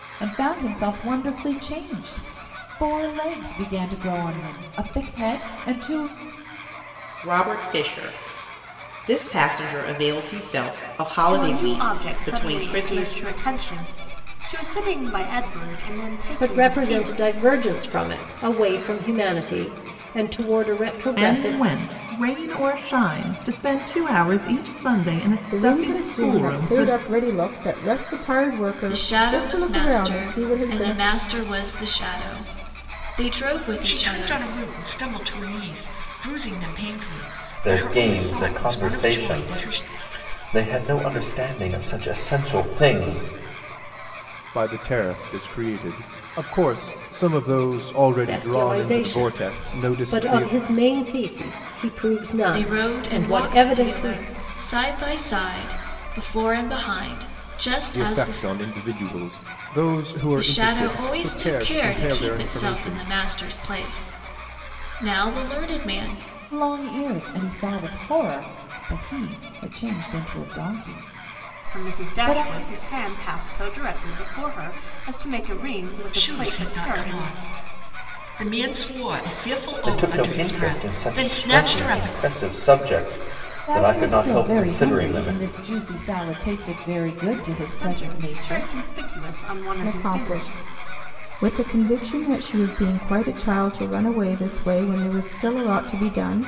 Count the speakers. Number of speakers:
ten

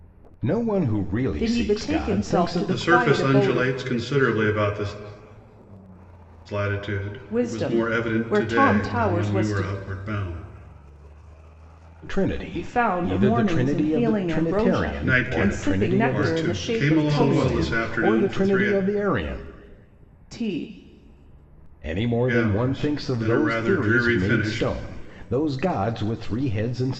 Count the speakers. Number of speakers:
three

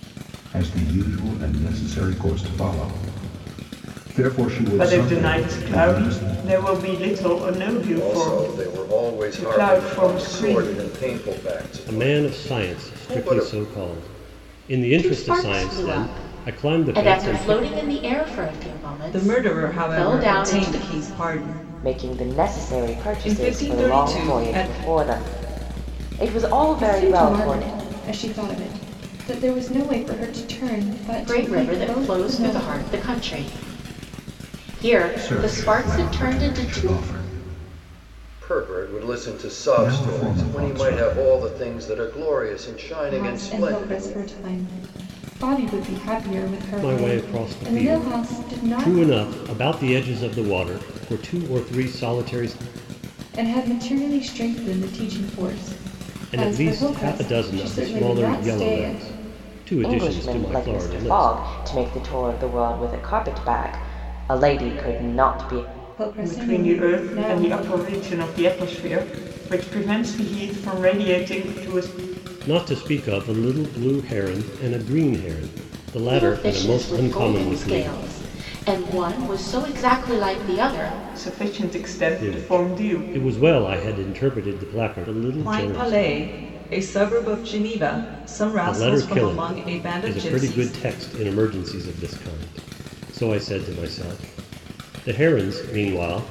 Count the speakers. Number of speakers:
eight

